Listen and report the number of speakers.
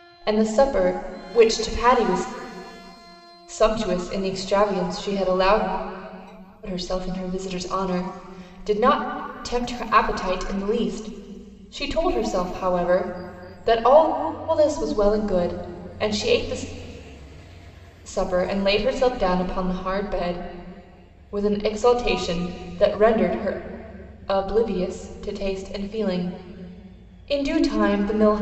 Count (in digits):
1